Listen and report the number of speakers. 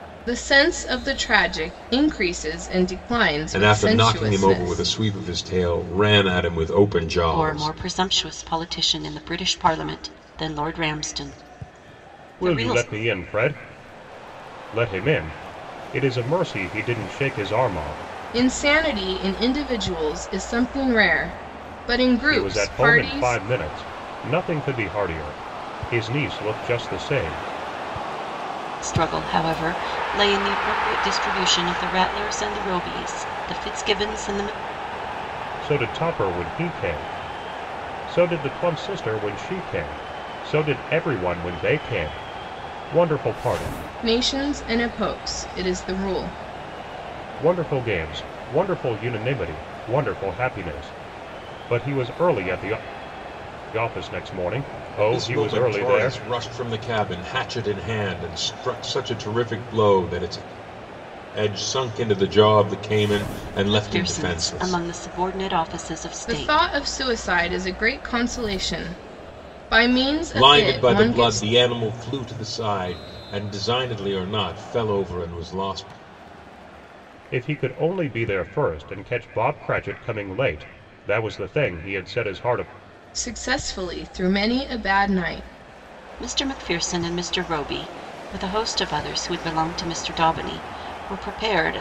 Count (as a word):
four